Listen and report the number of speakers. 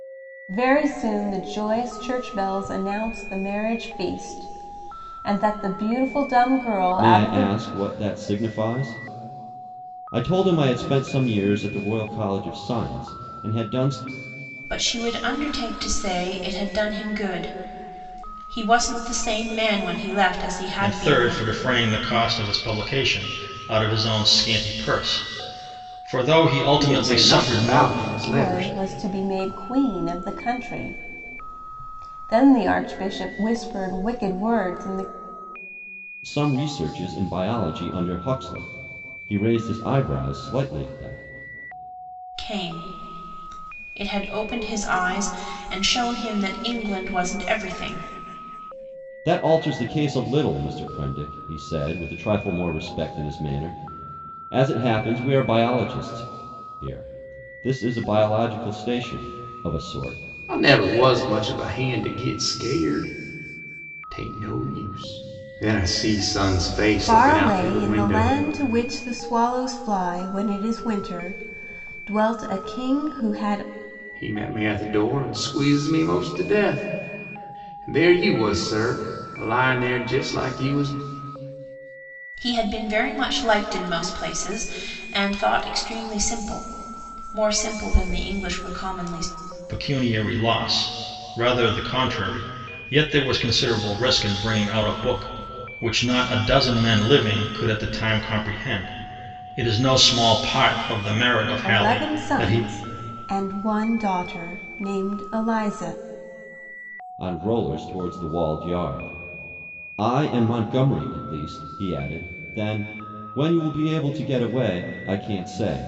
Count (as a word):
five